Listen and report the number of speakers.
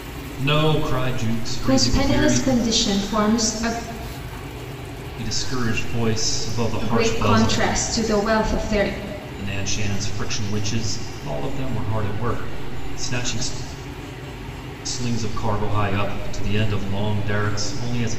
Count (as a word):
two